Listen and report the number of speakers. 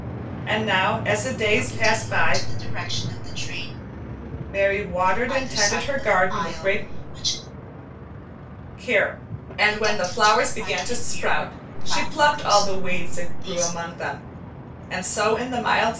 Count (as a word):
two